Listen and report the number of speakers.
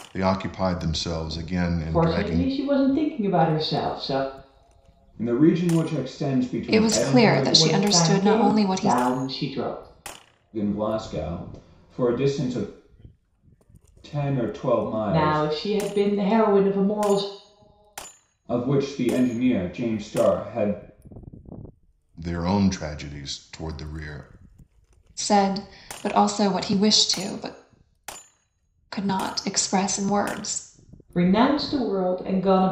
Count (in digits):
4